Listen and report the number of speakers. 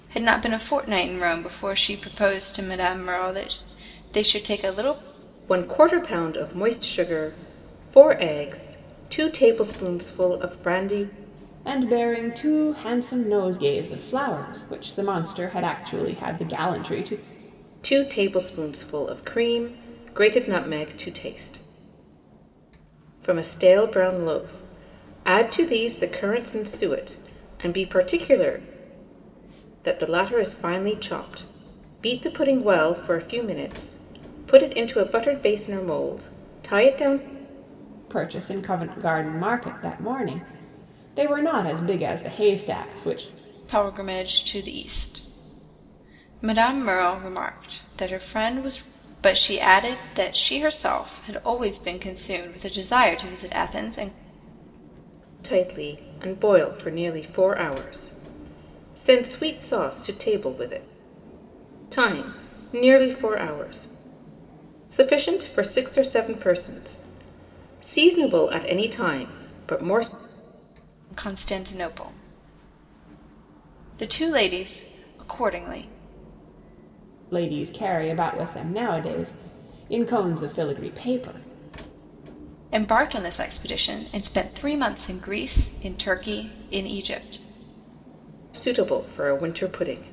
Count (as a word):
three